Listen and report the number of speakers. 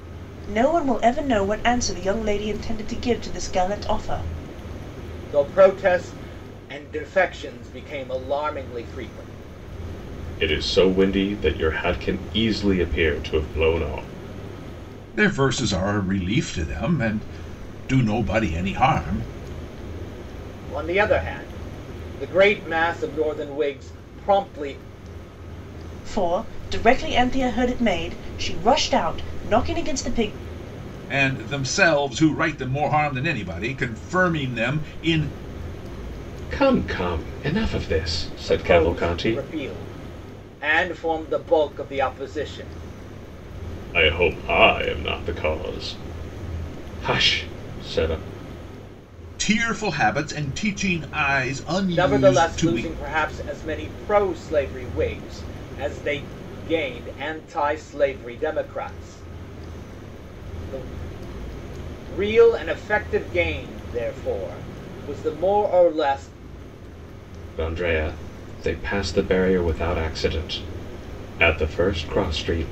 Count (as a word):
four